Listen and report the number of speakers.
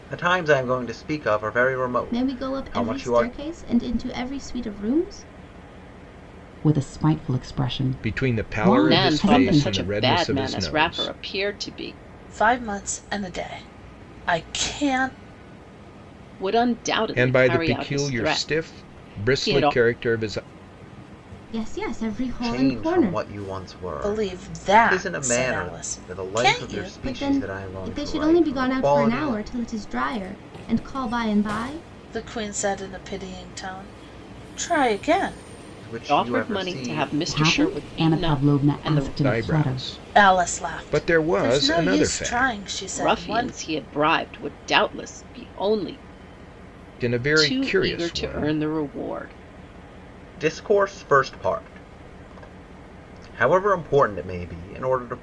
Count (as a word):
six